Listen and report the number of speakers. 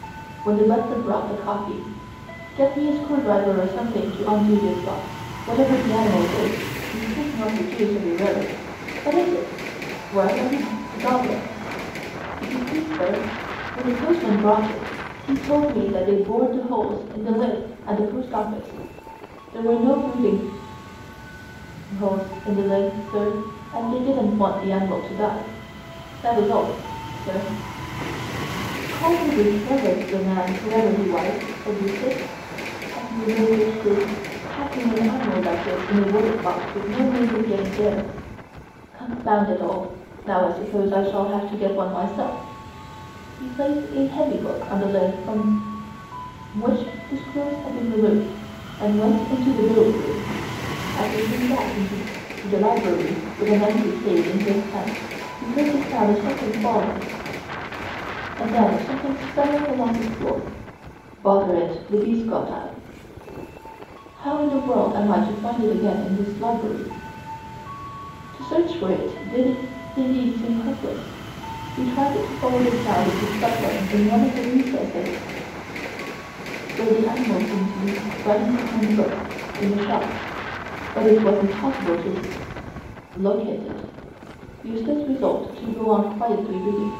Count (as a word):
one